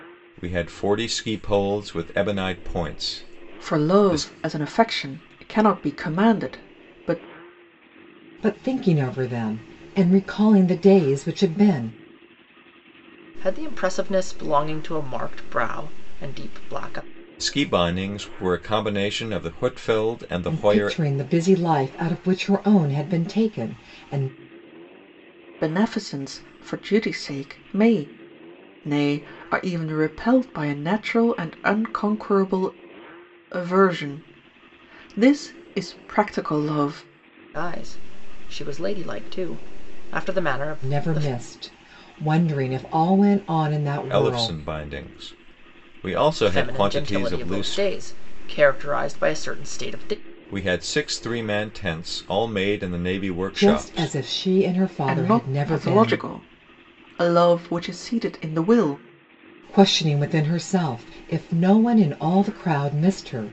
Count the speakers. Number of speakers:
4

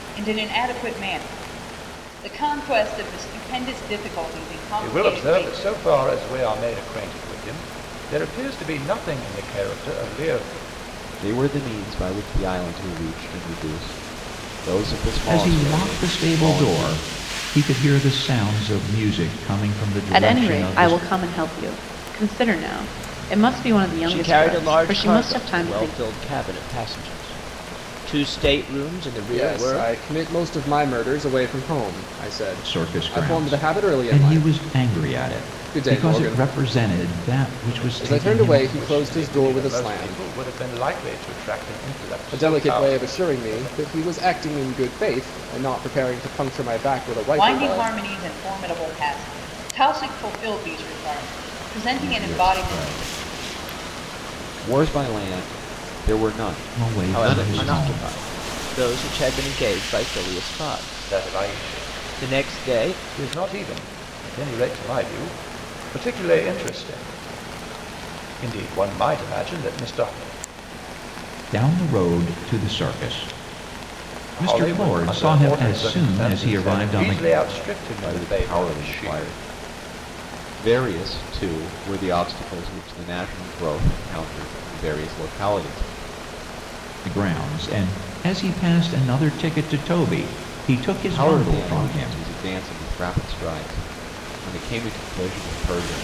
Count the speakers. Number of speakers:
7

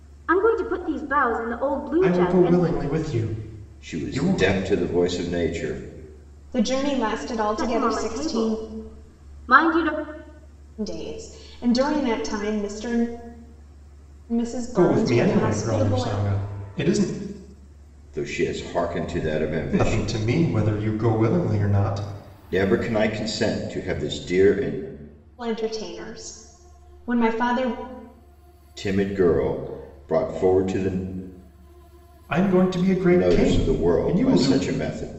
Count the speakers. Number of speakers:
4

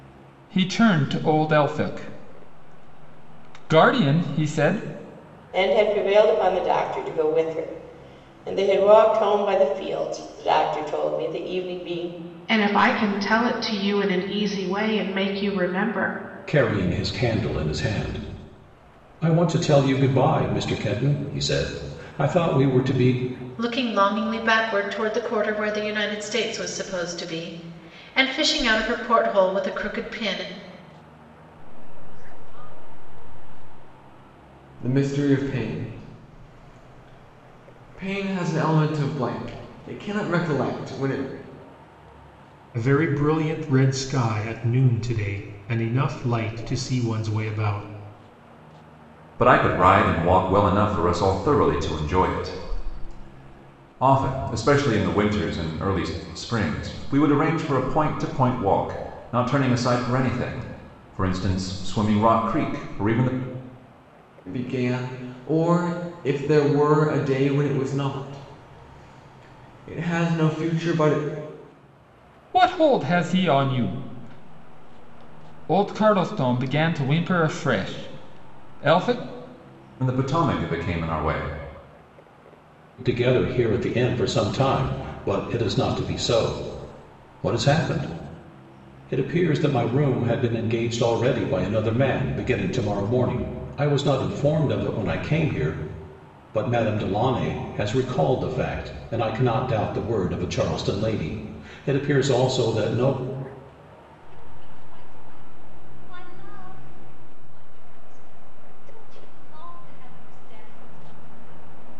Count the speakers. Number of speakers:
9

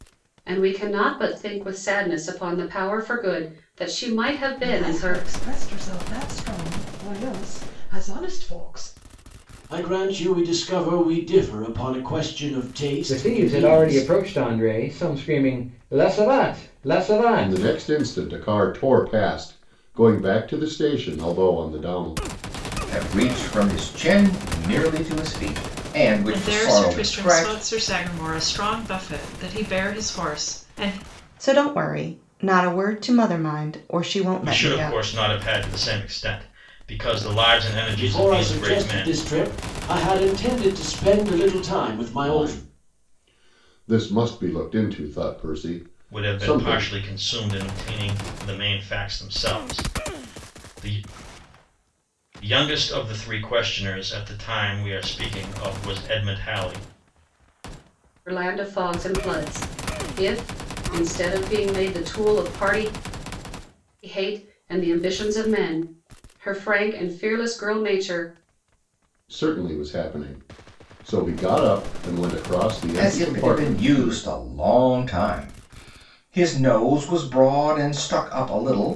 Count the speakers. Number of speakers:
9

